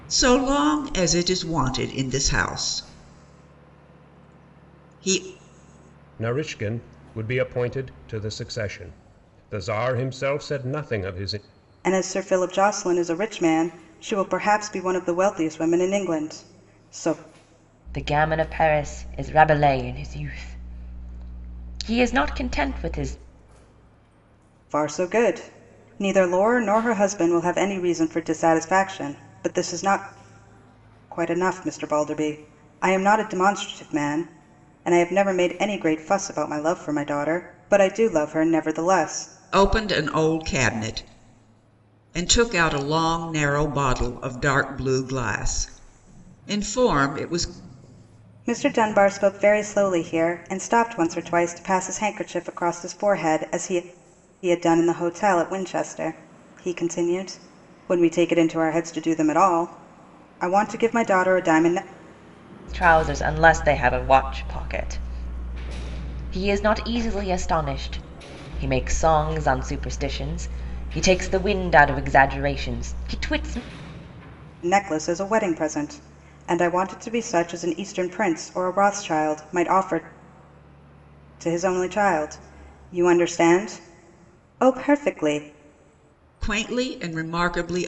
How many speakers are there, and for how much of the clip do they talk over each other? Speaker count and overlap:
4, no overlap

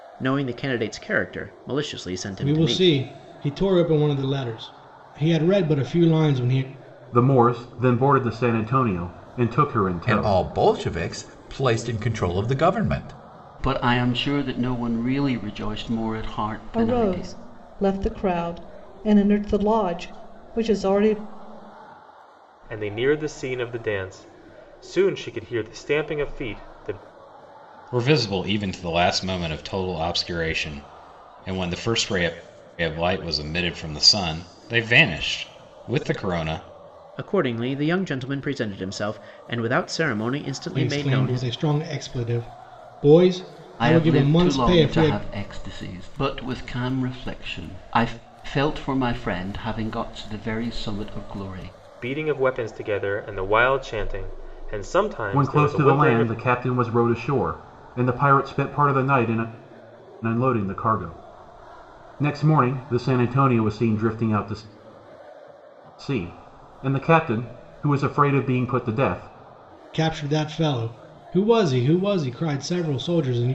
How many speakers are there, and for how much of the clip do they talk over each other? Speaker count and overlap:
8, about 7%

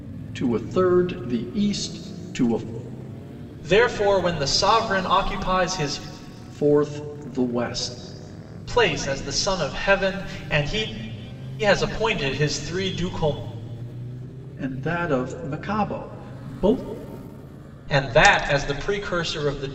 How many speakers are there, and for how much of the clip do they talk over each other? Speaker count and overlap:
2, no overlap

